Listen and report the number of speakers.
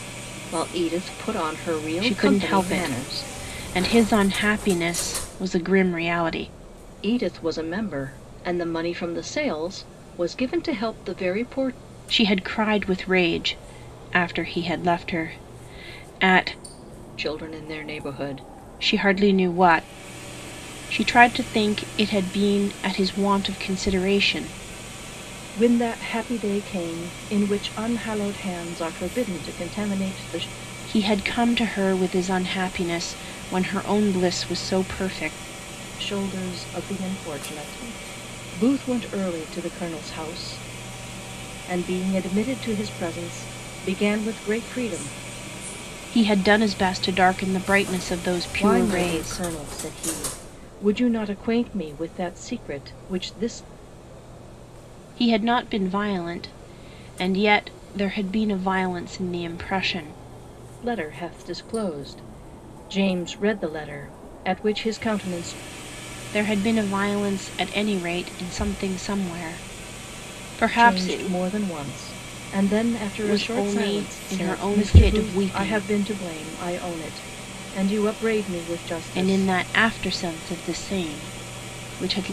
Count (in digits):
2